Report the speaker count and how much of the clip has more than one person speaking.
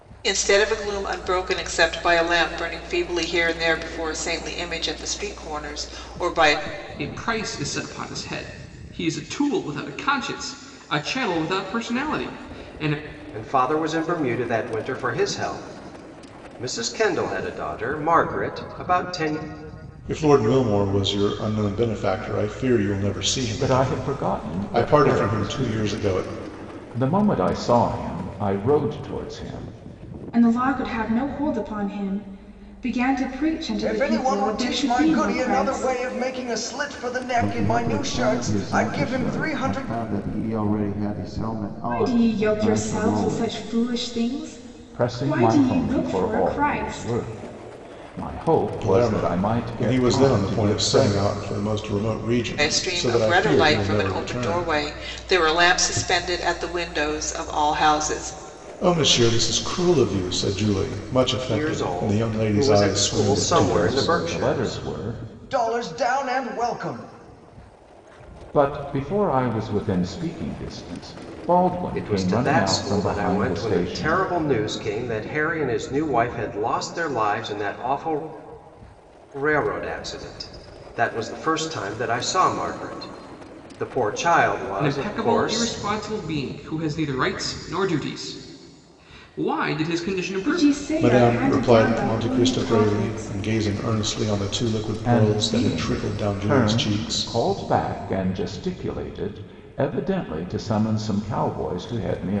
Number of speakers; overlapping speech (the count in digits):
8, about 27%